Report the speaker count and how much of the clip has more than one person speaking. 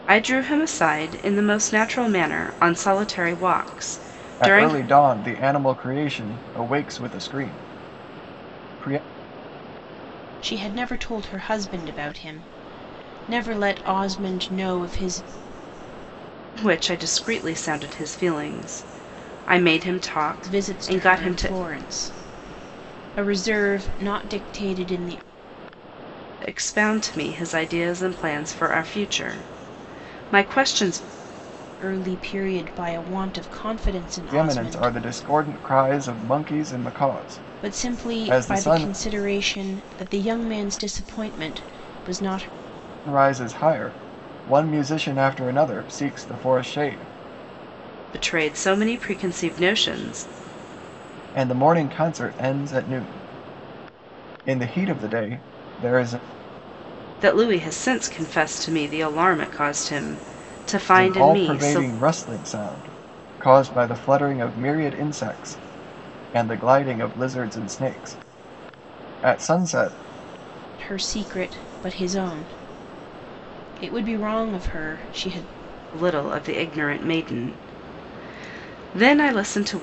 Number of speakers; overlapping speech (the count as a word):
three, about 6%